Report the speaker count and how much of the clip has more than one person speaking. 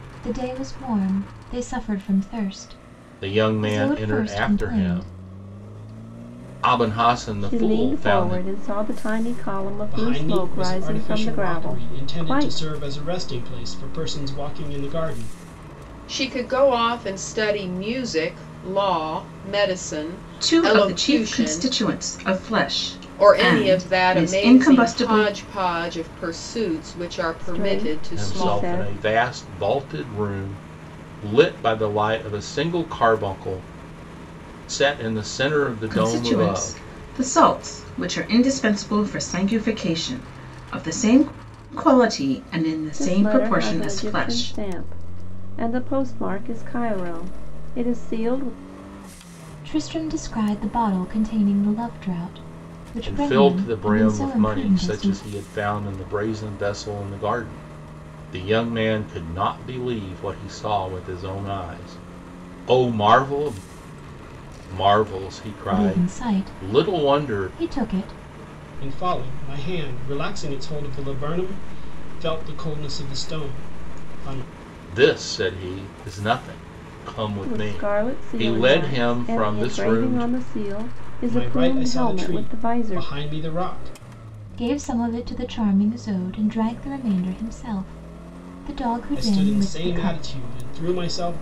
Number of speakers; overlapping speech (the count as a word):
six, about 26%